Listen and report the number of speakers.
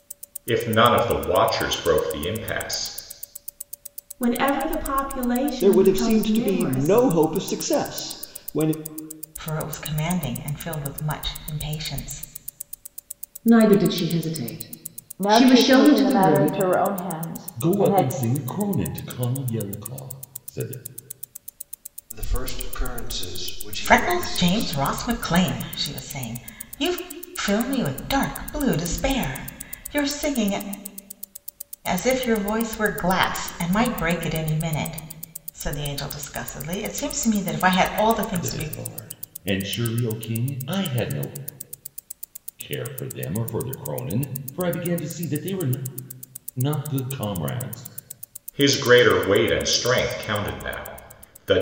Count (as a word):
eight